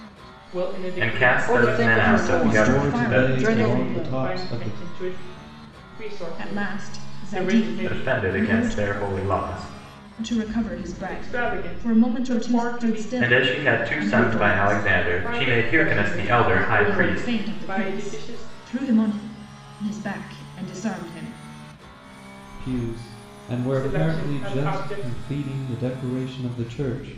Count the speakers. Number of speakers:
five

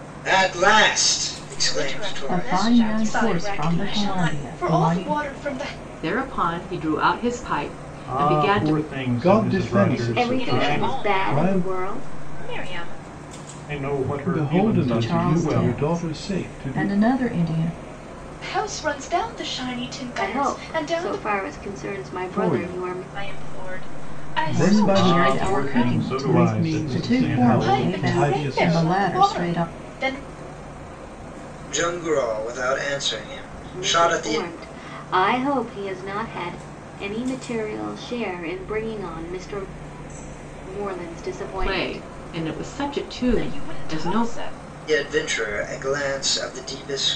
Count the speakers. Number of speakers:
eight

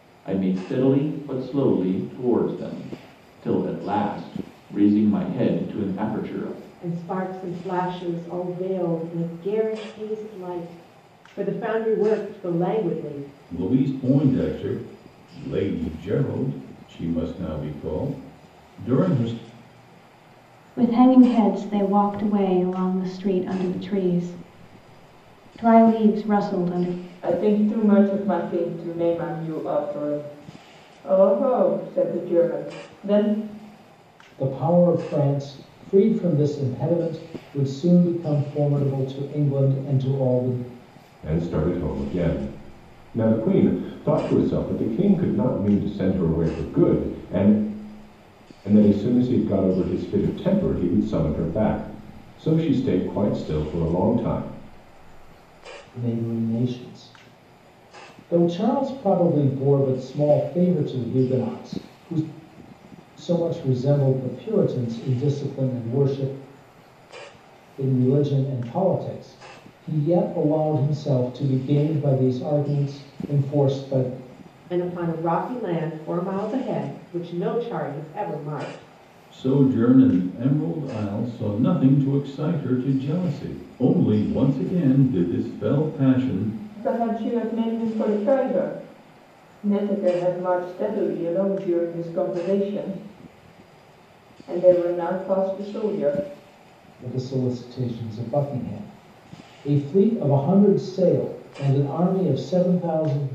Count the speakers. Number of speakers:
seven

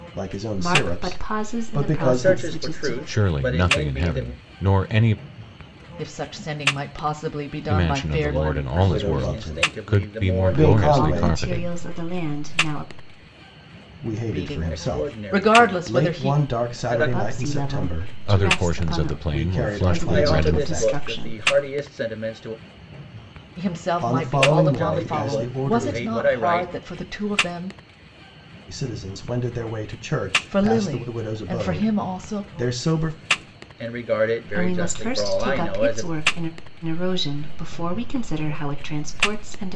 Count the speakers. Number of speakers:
five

